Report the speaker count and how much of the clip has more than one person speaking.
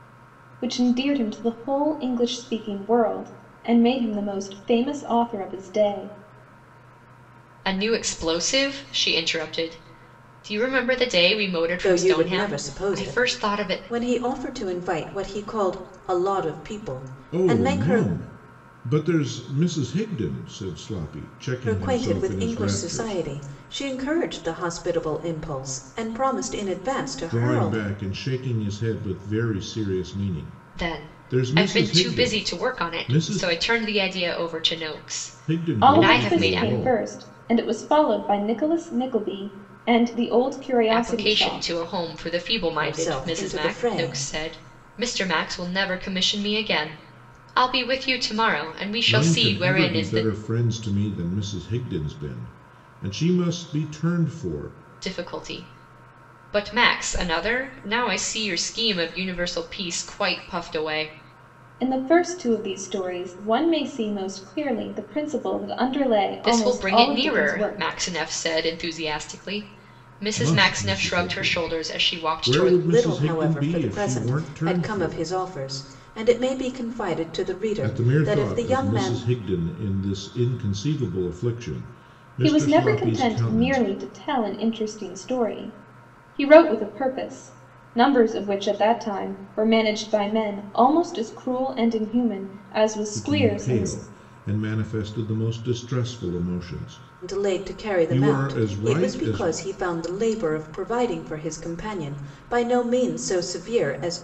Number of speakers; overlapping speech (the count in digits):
4, about 25%